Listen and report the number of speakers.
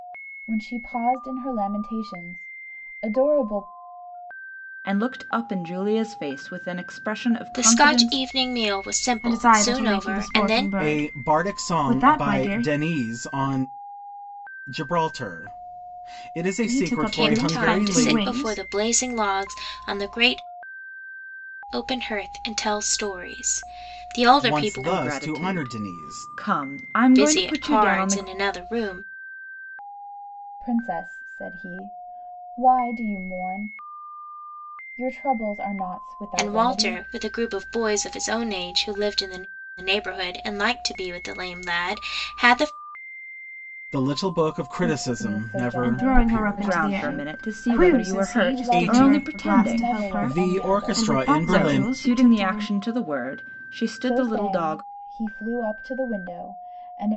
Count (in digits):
5